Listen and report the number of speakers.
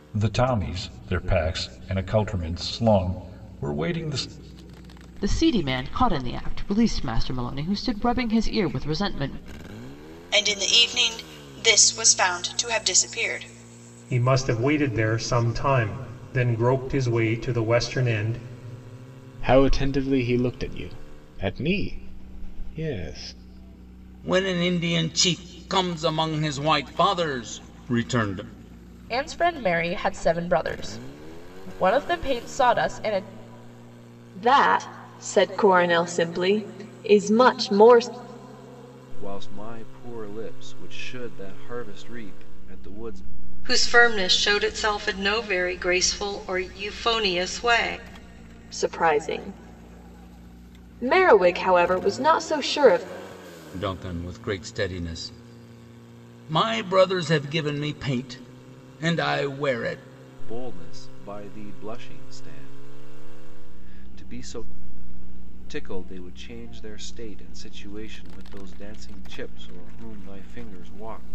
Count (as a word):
ten